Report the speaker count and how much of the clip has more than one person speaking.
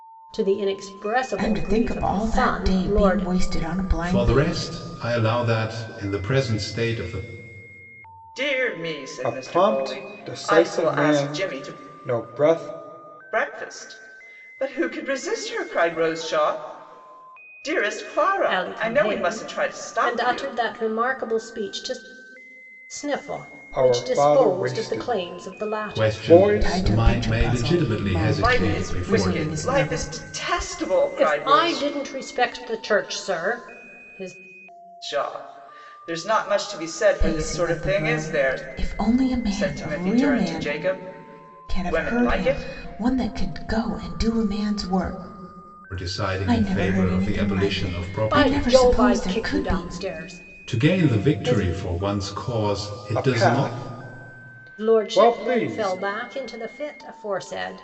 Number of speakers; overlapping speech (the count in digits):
5, about 42%